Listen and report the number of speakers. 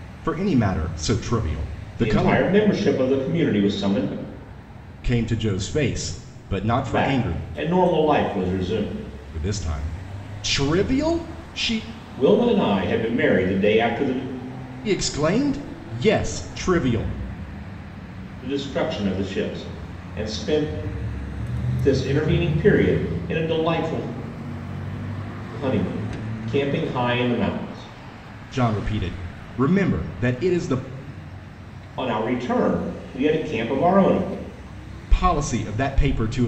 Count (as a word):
two